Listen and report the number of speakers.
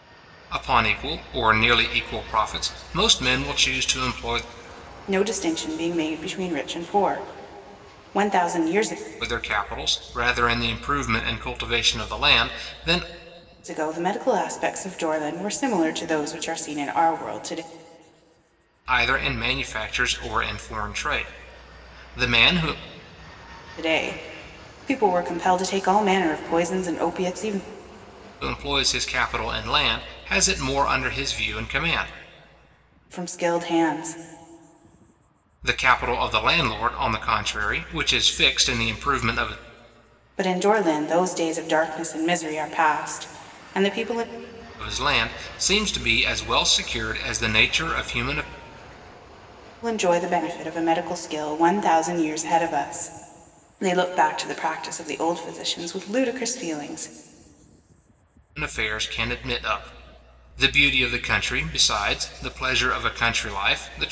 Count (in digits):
2